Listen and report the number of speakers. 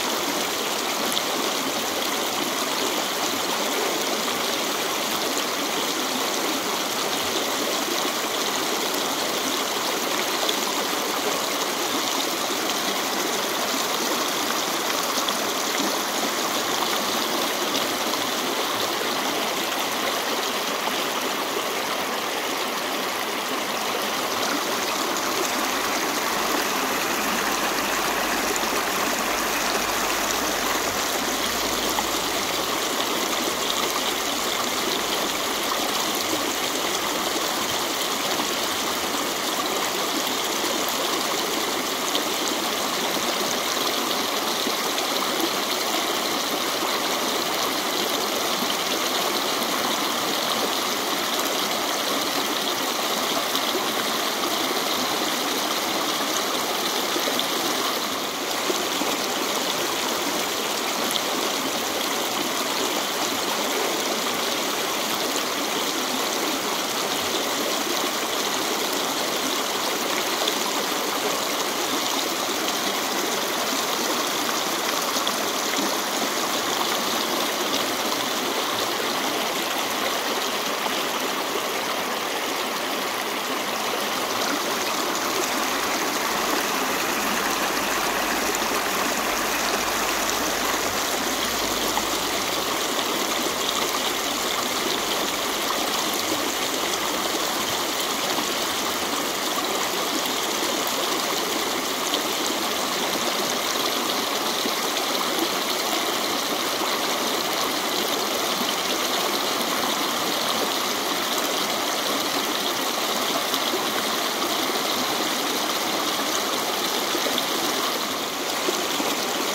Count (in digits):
0